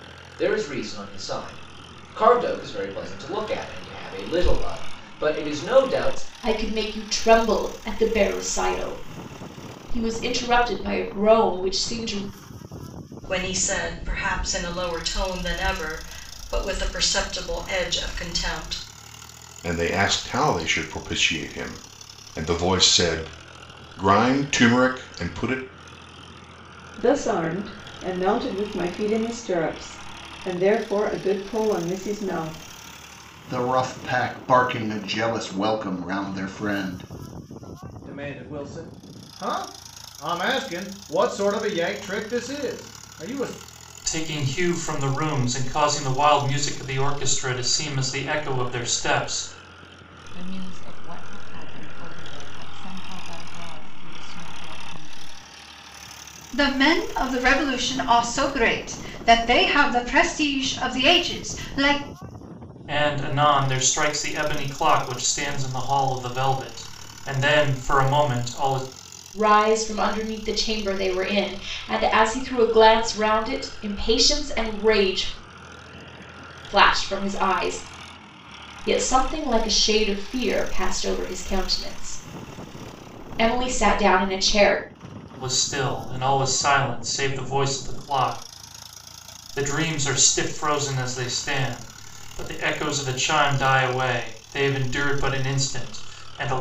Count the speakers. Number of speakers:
10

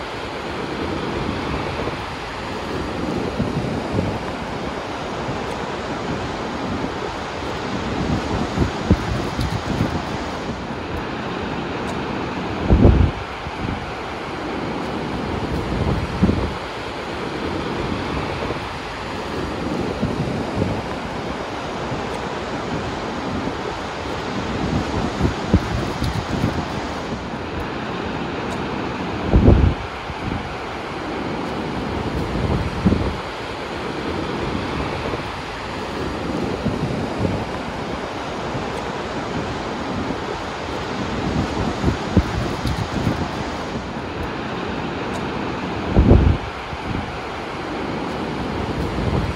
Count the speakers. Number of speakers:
0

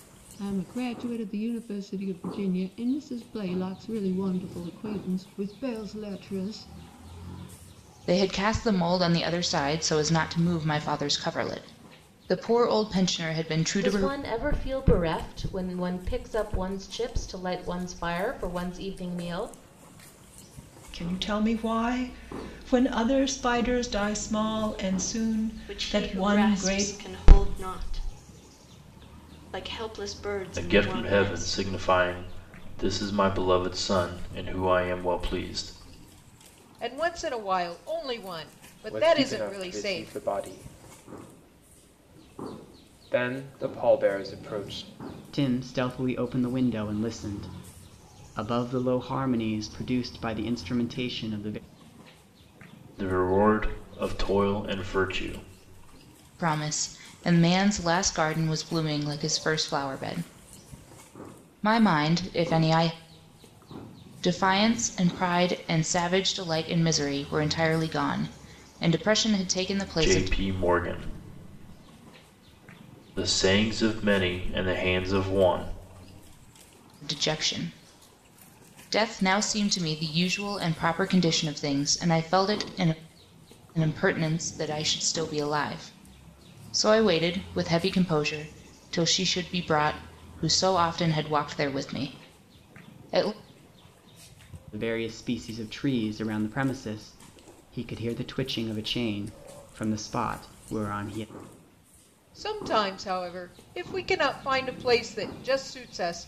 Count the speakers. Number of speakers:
9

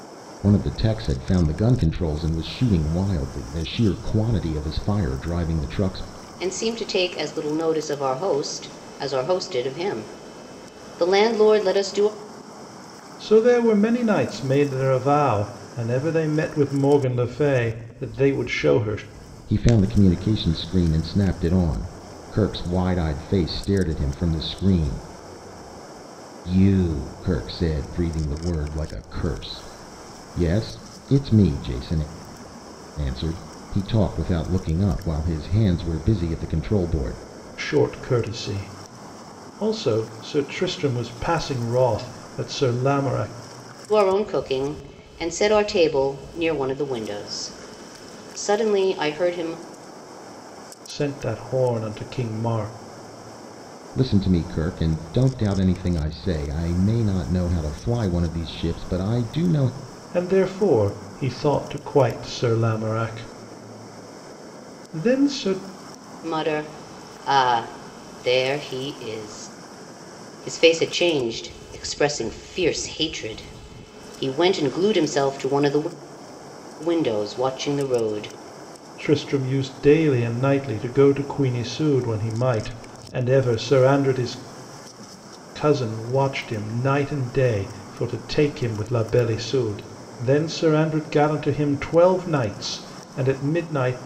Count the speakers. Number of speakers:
3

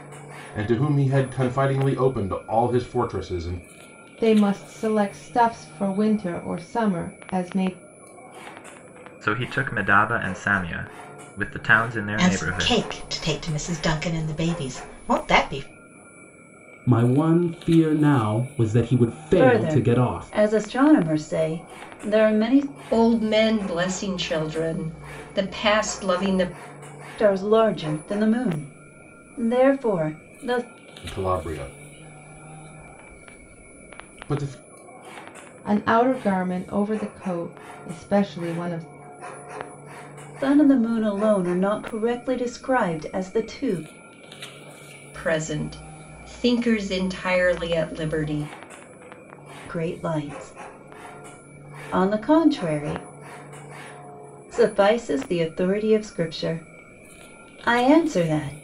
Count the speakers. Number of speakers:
7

